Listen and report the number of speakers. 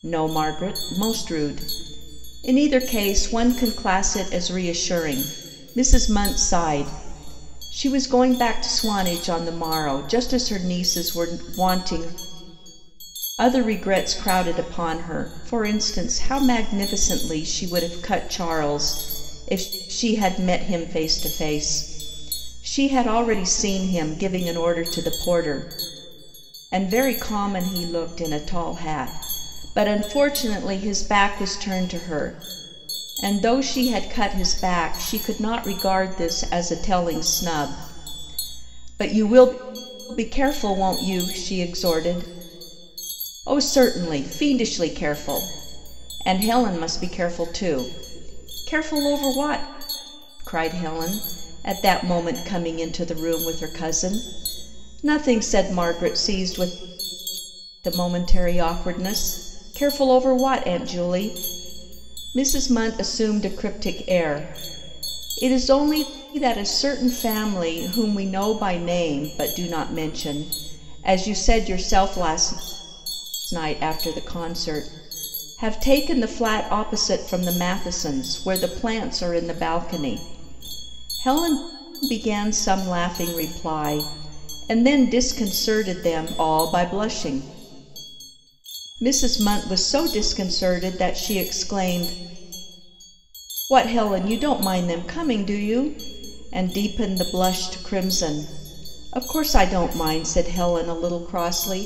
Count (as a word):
one